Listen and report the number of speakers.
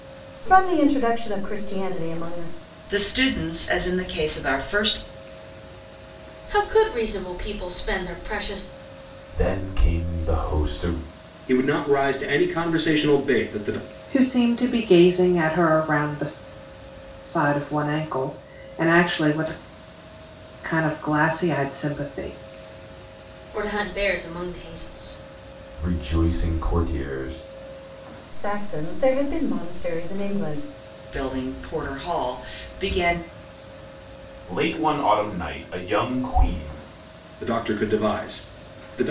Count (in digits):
6